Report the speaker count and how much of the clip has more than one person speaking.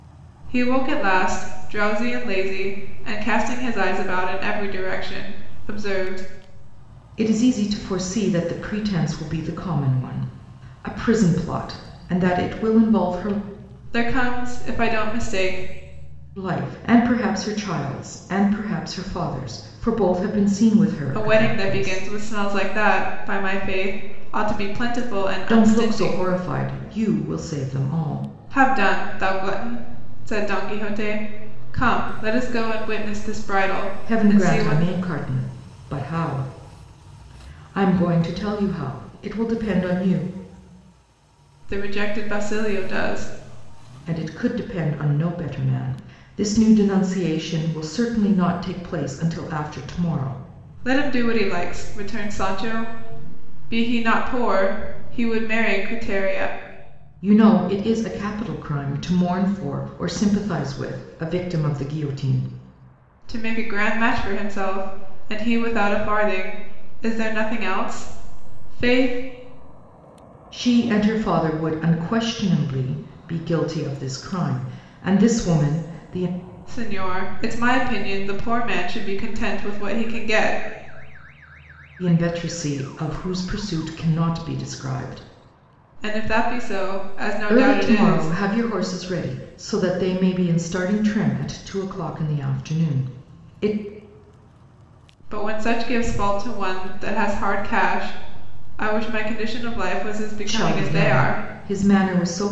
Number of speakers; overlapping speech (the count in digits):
2, about 4%